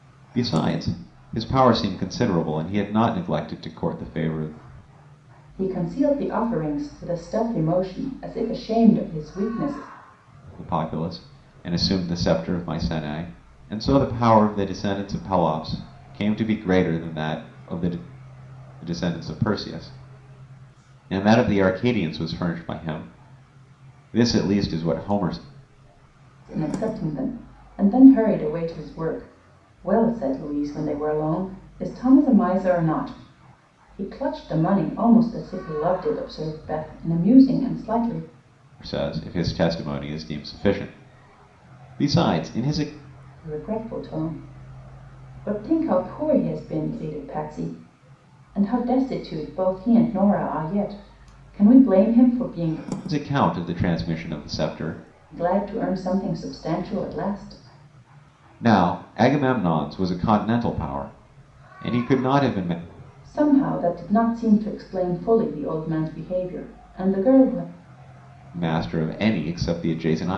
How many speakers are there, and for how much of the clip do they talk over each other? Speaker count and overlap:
2, no overlap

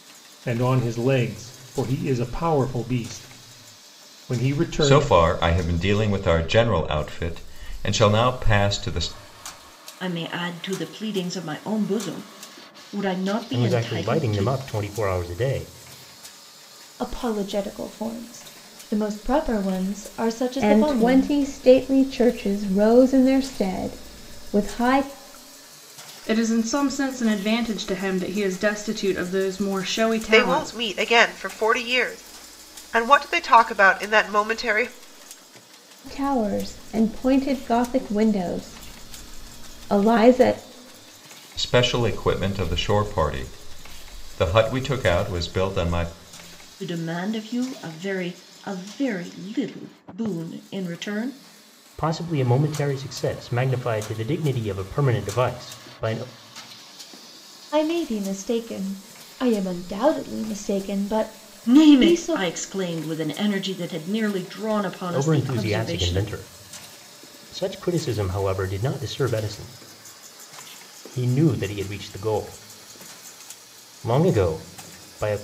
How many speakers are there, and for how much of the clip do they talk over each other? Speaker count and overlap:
8, about 6%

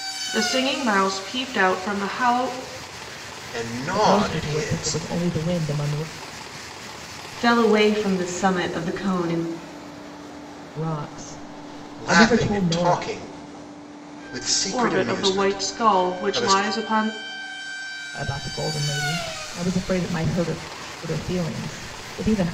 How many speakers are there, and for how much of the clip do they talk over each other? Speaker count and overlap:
4, about 18%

